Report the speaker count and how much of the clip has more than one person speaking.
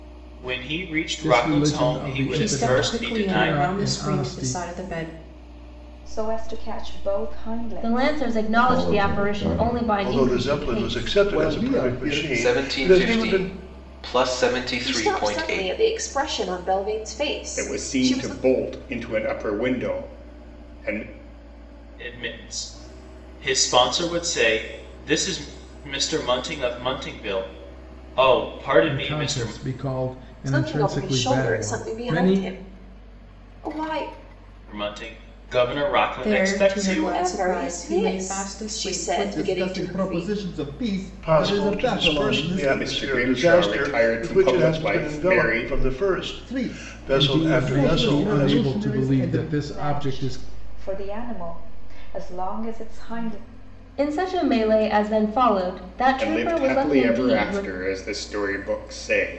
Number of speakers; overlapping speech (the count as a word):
ten, about 47%